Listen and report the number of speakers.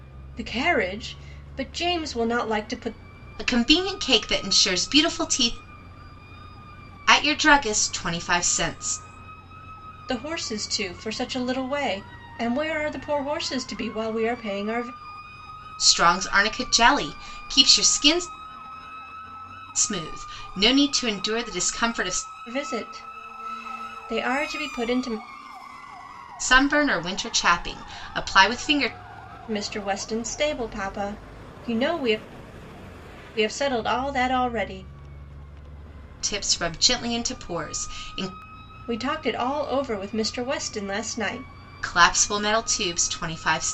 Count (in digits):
2